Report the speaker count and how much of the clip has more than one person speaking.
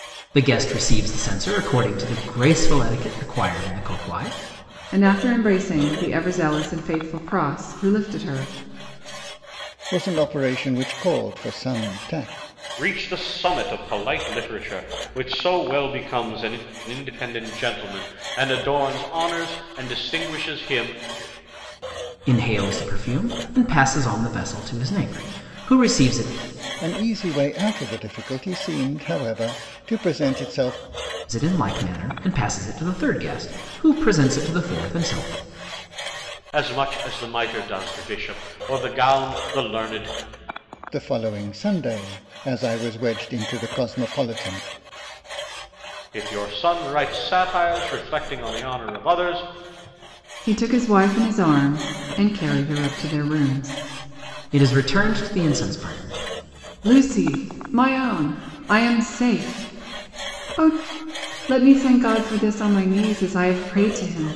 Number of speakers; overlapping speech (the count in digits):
4, no overlap